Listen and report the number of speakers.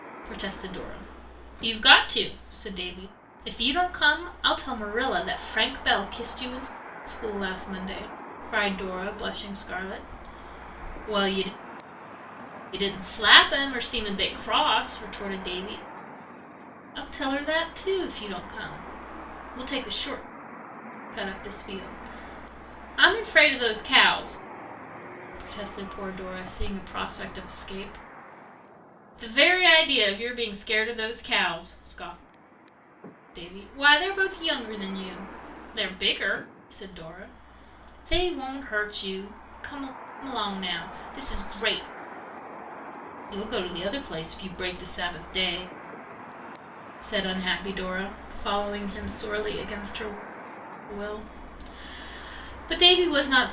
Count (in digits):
1